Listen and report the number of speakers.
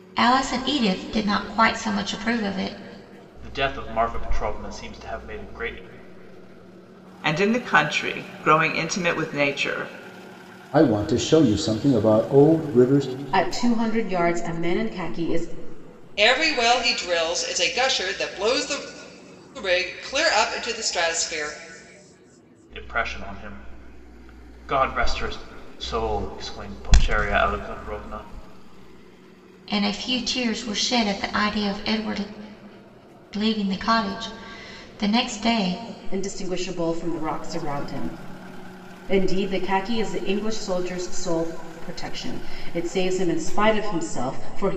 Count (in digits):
6